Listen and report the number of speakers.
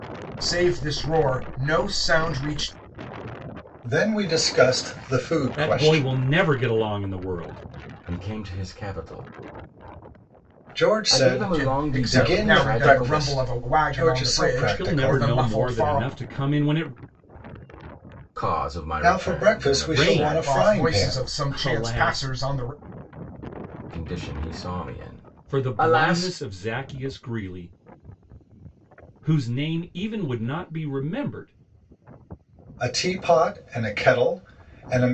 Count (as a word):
four